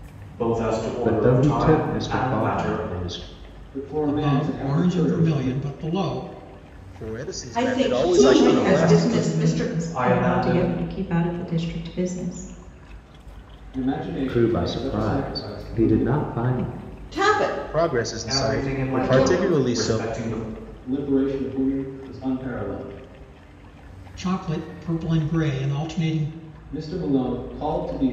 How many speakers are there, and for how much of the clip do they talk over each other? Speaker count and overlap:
7, about 38%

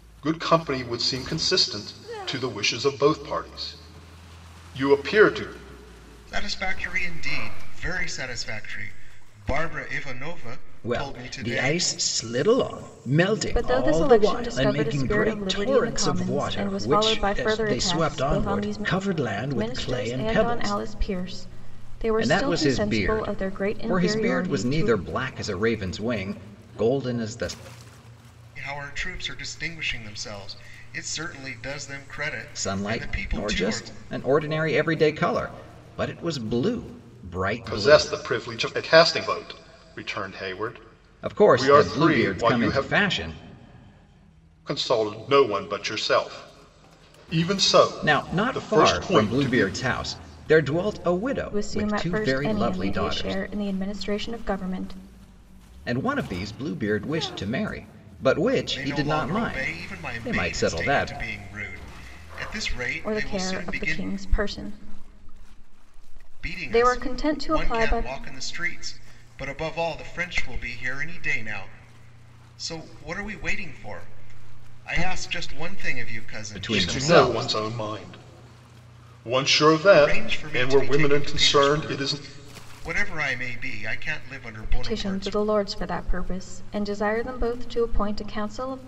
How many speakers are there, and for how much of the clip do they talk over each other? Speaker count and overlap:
4, about 31%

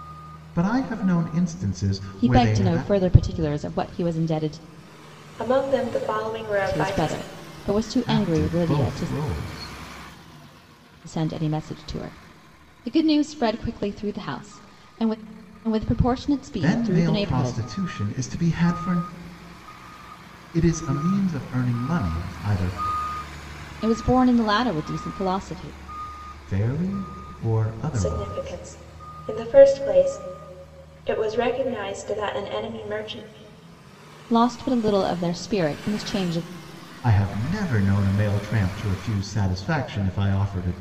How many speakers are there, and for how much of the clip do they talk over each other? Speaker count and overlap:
3, about 10%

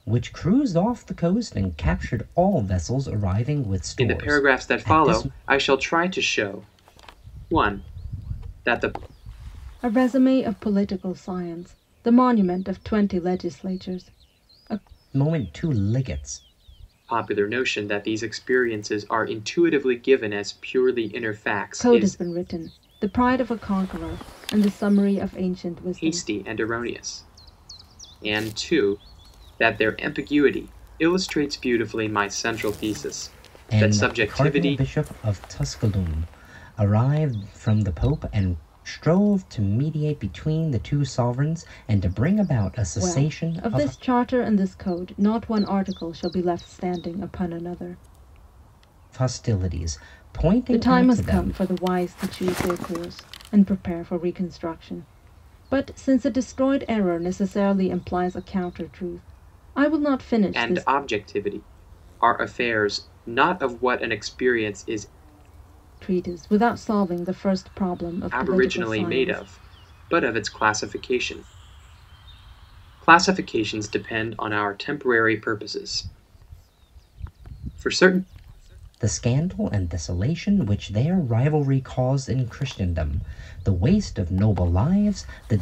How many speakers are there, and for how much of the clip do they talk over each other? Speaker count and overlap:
3, about 8%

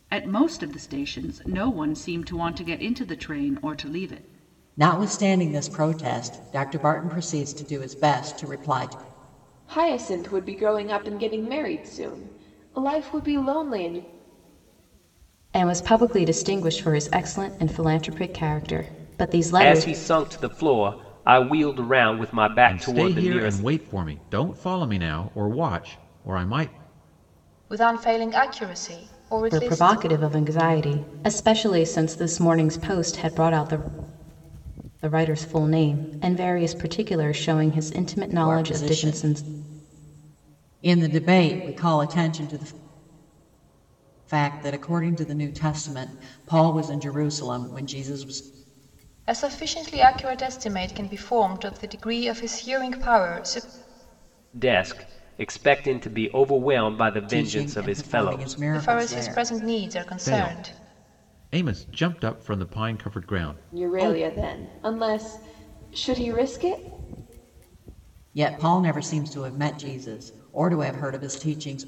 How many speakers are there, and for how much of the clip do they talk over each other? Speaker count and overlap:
7, about 9%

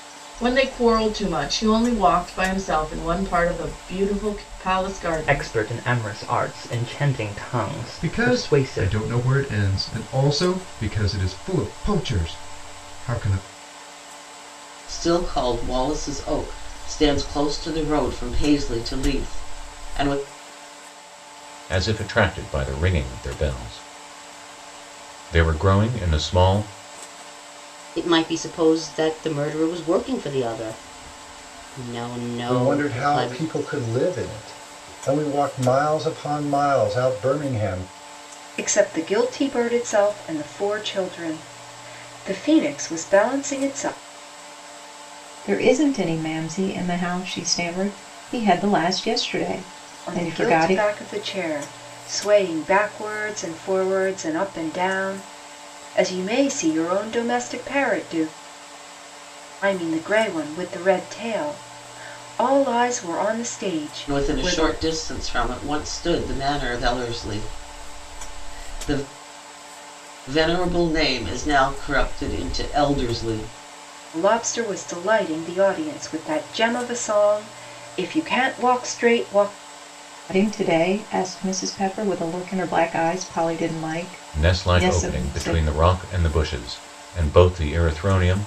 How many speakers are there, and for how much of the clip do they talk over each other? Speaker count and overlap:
9, about 6%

